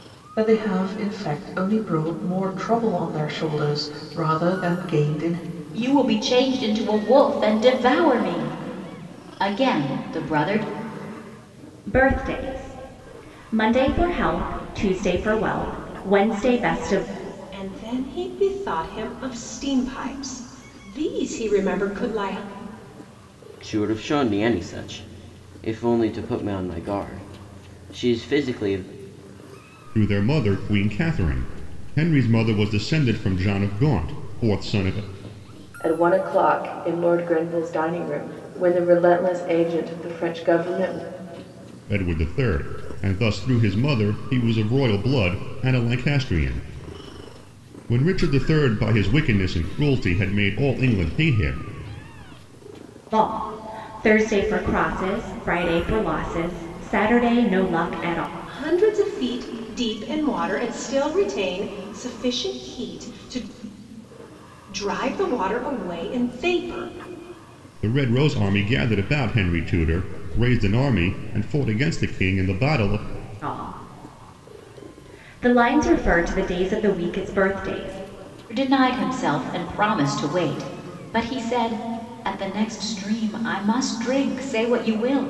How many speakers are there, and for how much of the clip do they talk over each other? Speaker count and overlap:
7, no overlap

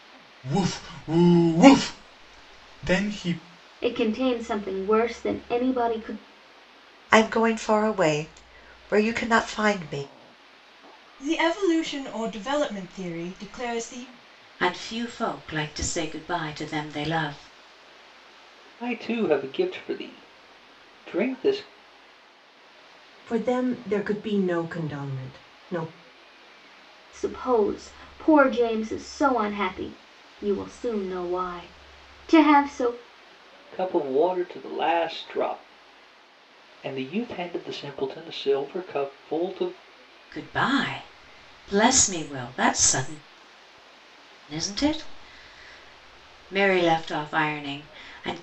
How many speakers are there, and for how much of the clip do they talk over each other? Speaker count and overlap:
7, no overlap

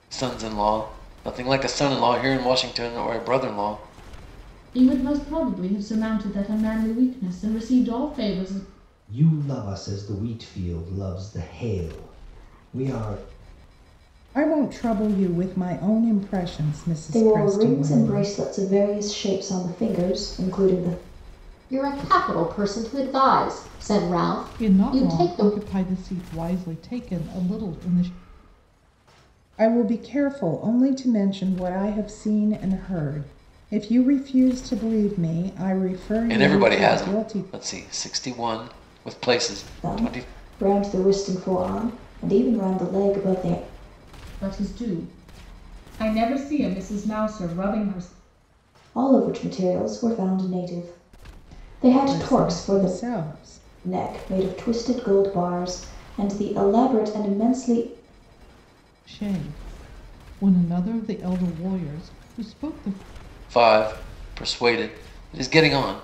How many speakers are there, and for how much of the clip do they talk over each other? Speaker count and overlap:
7, about 8%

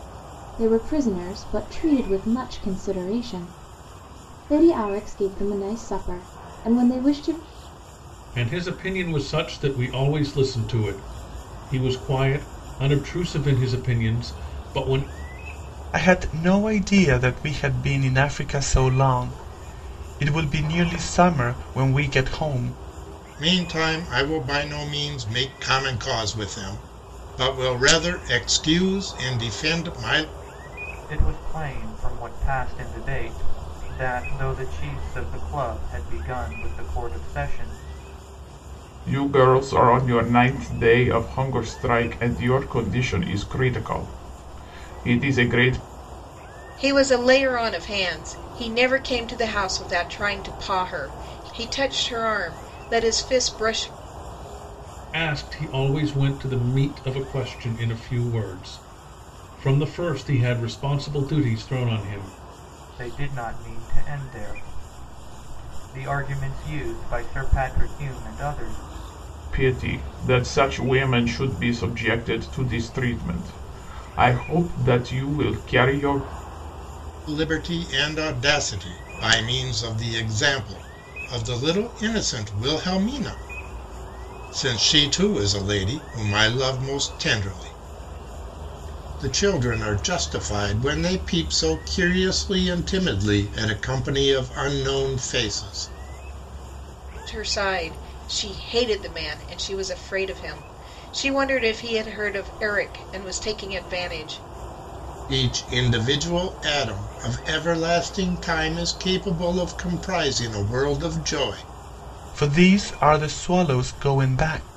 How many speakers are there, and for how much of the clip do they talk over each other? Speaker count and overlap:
7, no overlap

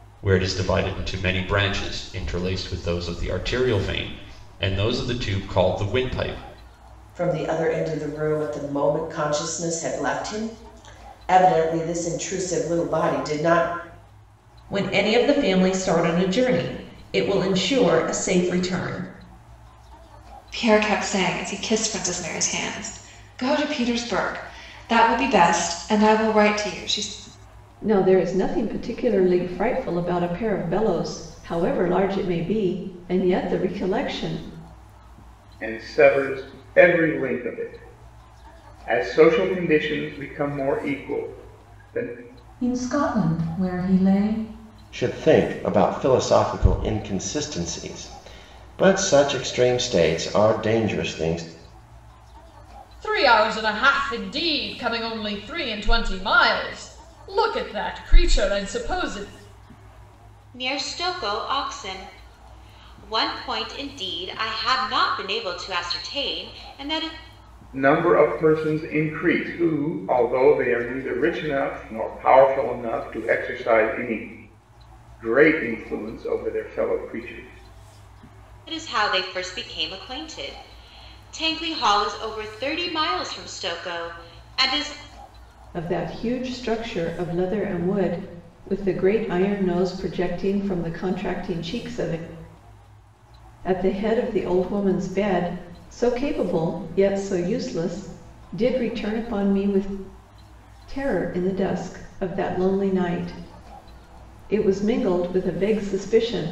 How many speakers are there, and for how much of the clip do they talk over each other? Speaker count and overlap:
10, no overlap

